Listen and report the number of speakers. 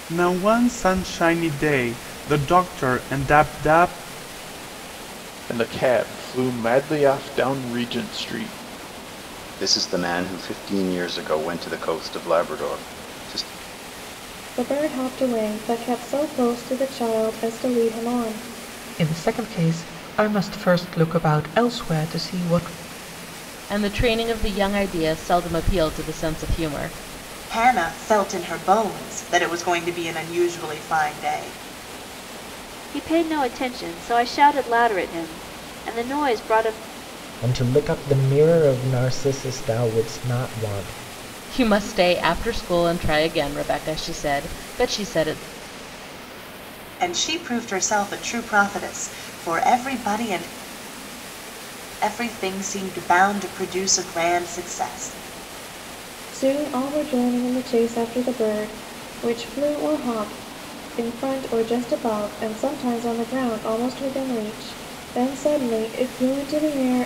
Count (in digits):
9